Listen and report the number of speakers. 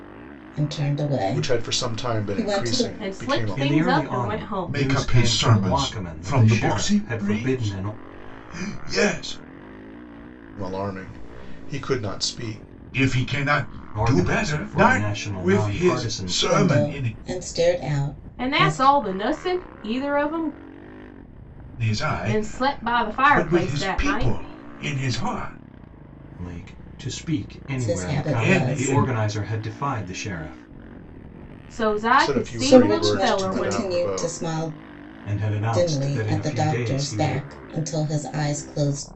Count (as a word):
five